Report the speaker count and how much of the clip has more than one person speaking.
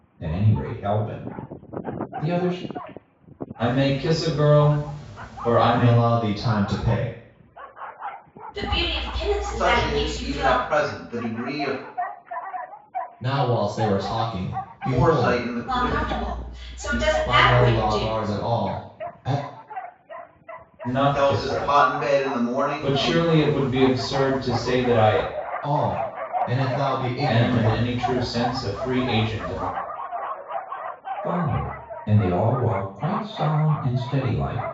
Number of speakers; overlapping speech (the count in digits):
5, about 17%